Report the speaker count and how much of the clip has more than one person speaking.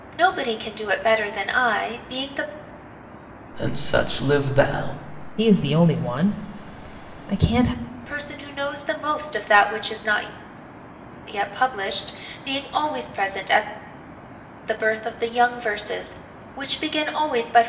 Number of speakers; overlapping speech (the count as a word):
three, no overlap